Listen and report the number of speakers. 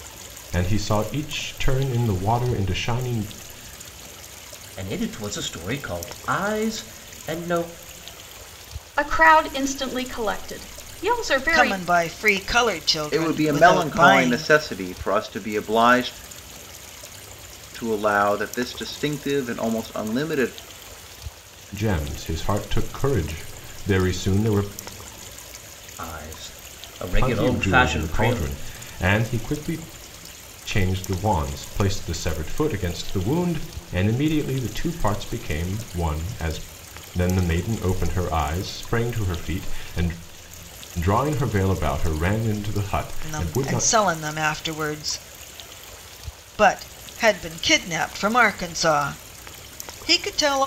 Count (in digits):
5